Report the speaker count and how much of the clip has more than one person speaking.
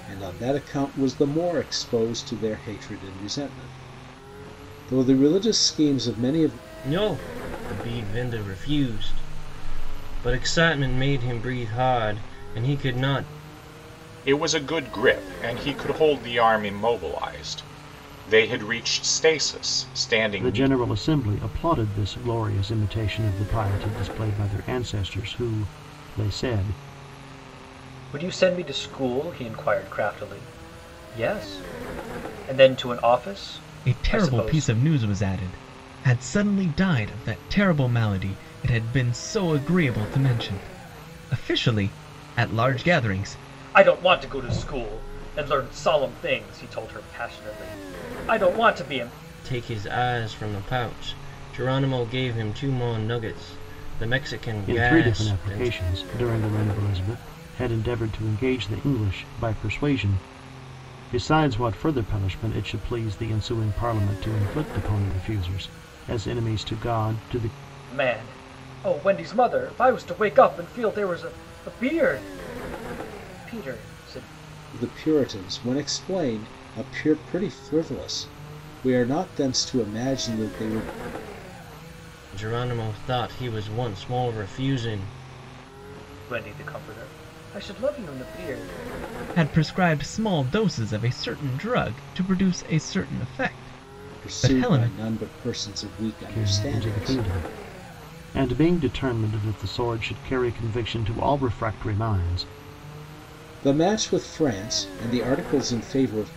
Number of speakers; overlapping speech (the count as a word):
six, about 5%